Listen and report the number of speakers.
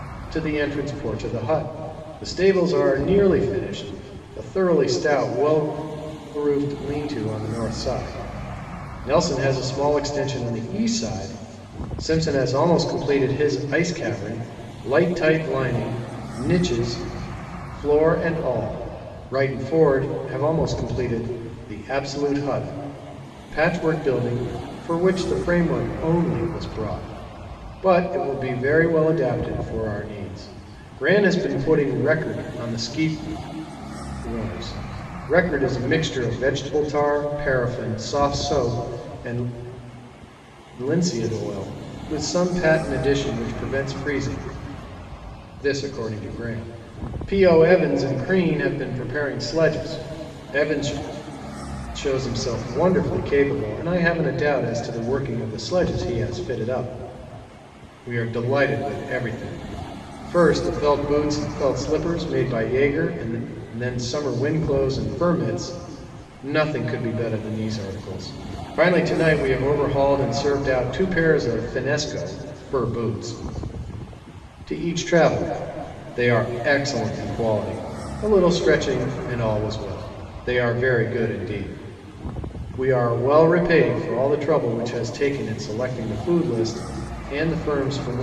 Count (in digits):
1